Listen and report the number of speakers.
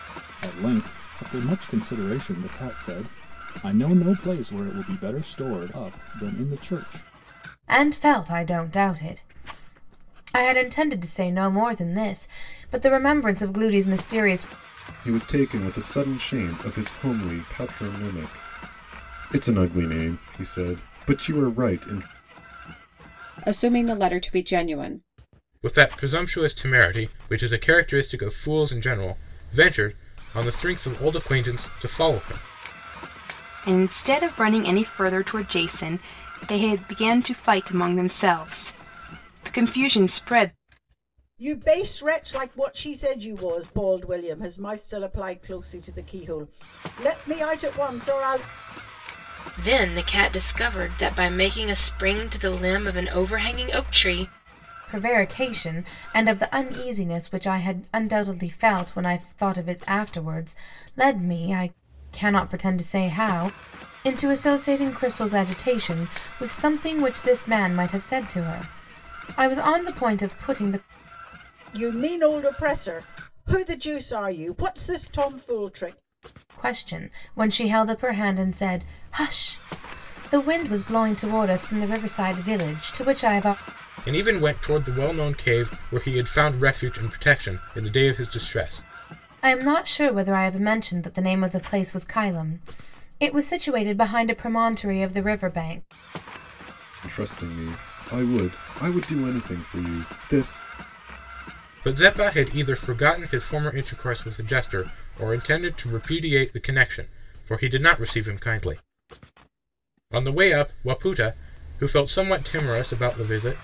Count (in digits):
8